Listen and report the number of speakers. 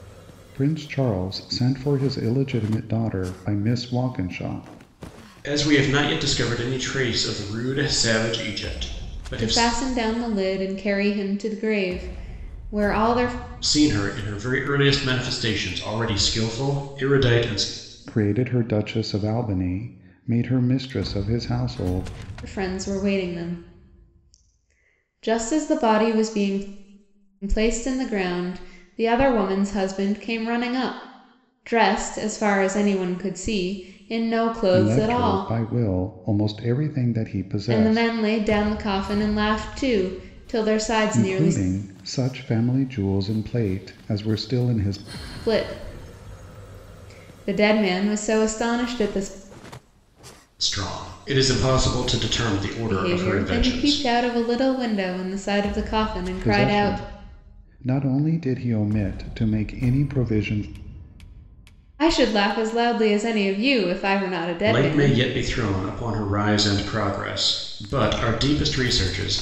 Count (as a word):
three